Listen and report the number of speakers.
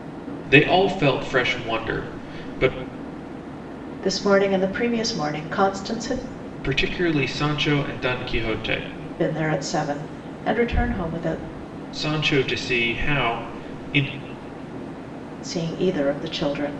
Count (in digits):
2